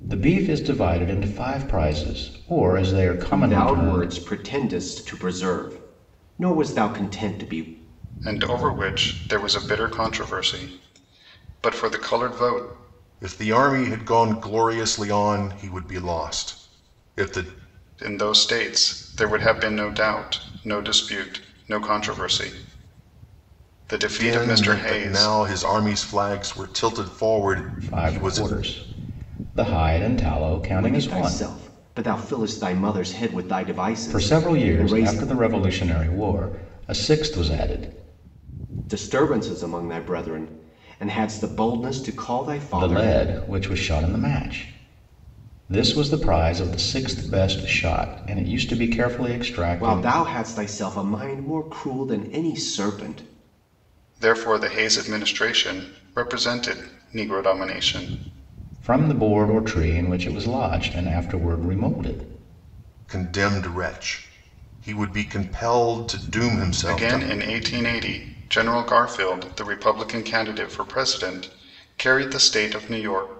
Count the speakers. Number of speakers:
four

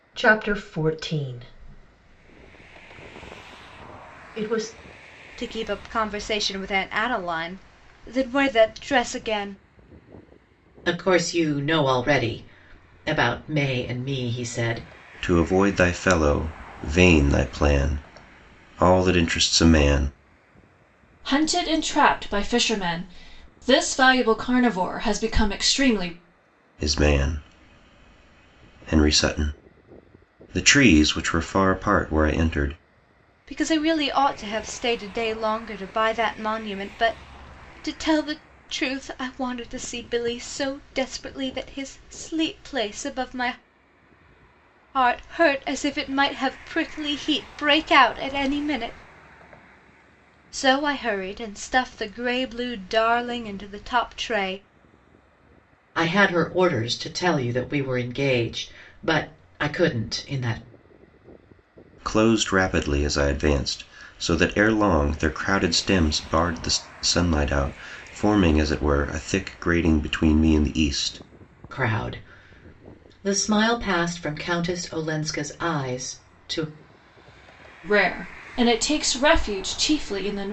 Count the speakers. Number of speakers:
five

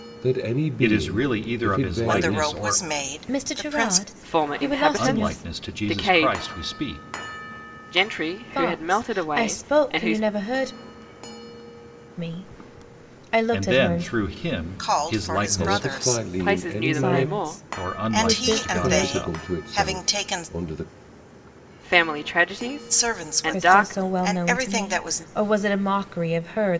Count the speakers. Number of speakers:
five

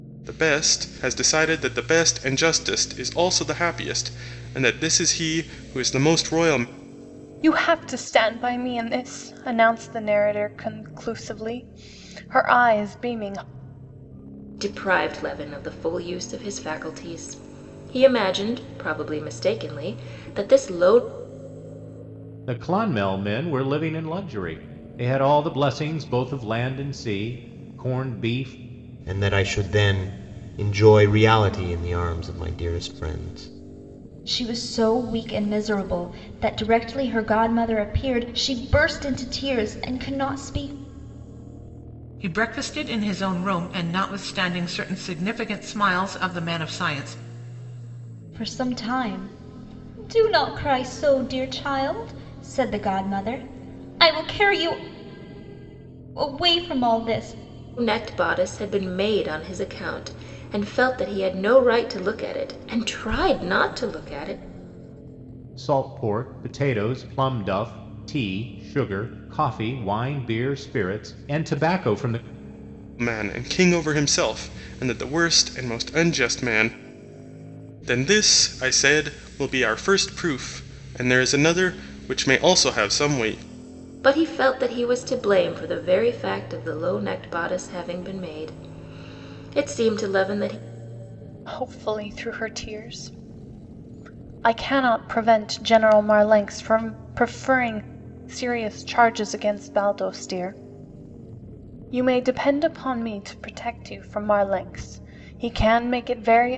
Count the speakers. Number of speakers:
seven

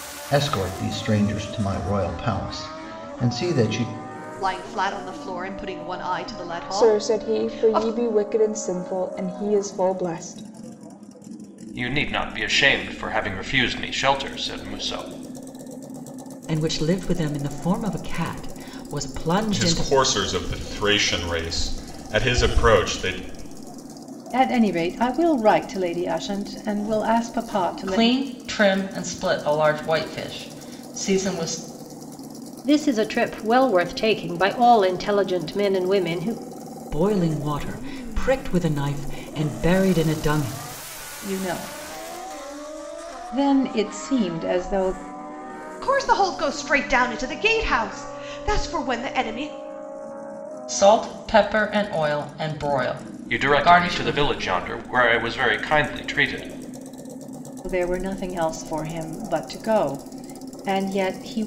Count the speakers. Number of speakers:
nine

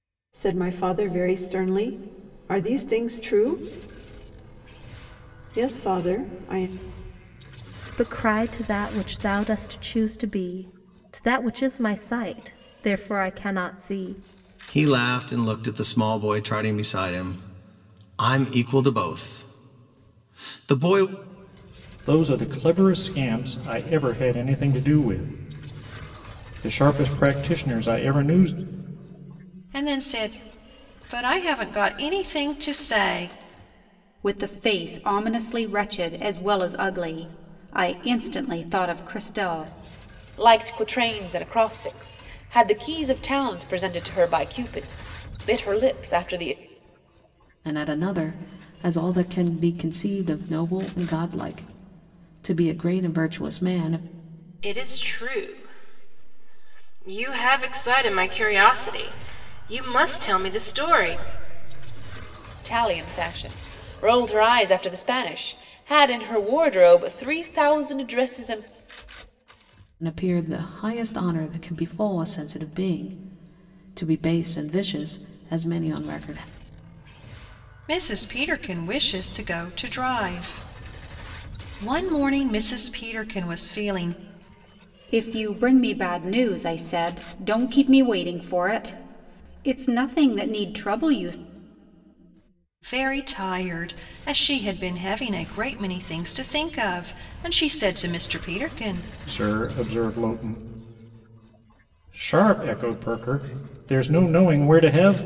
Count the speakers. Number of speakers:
nine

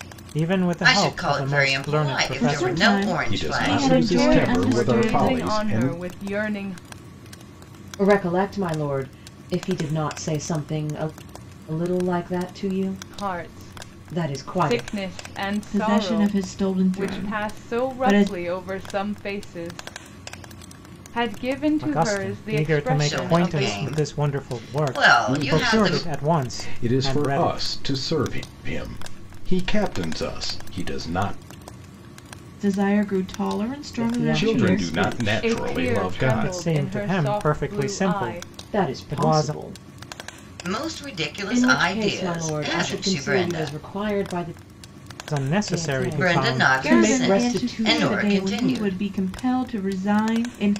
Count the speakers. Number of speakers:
six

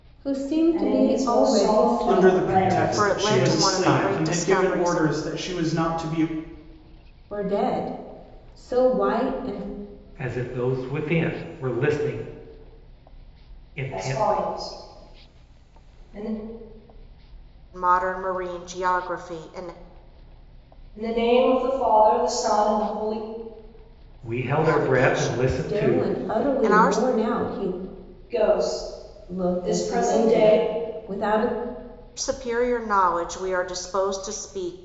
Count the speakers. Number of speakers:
five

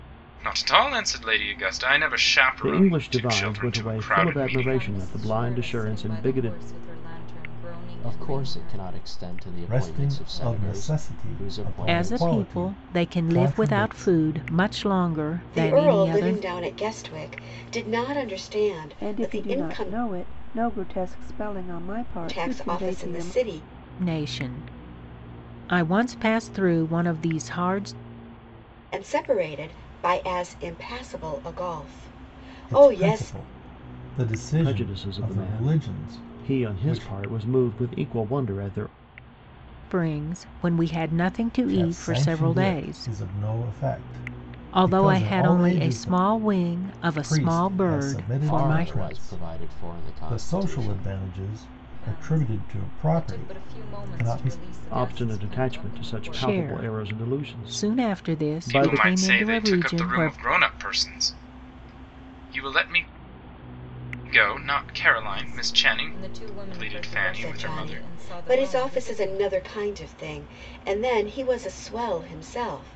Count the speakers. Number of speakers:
eight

